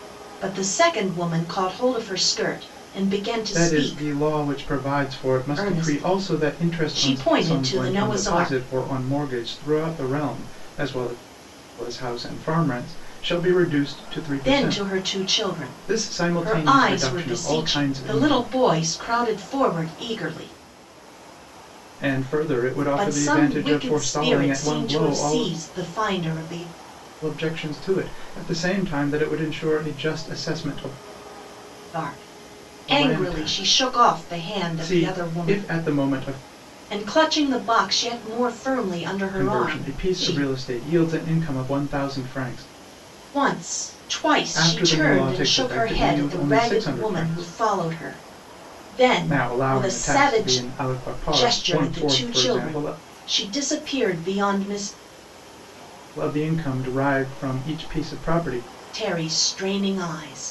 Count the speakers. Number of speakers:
2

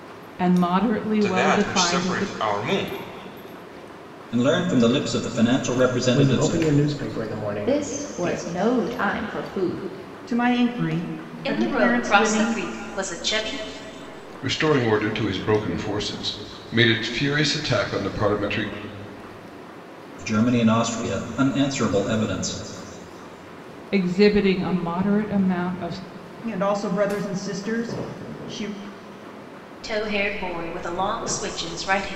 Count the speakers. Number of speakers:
8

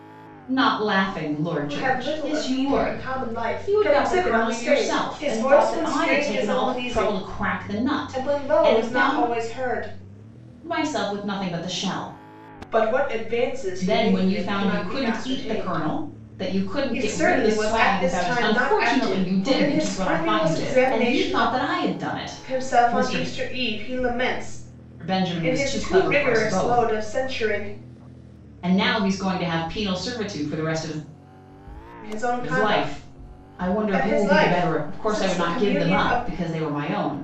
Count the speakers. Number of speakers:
2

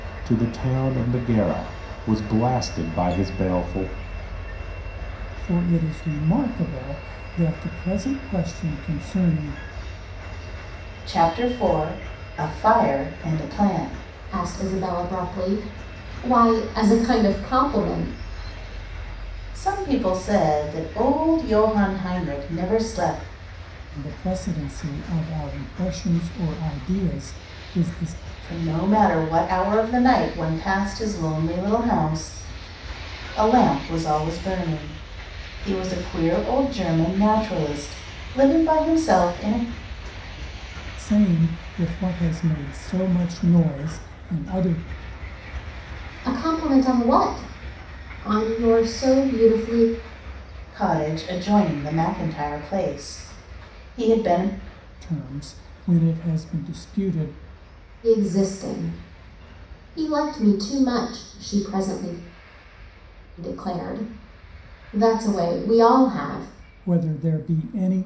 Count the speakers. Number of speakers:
4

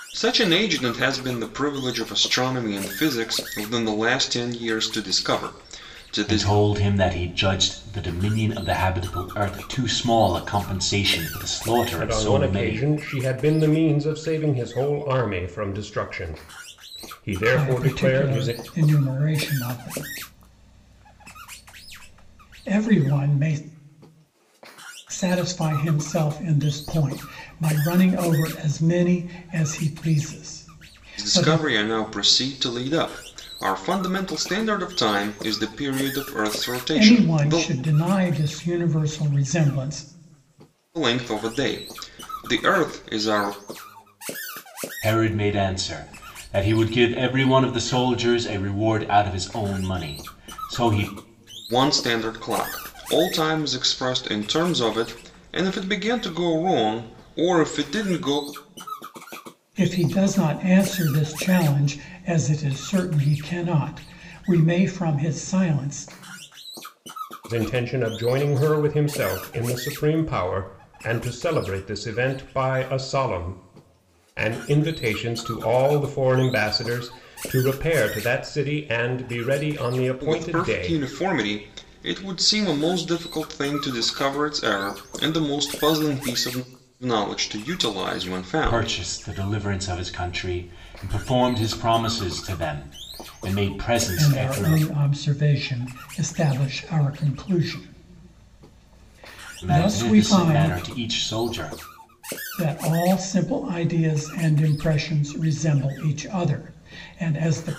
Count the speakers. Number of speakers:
4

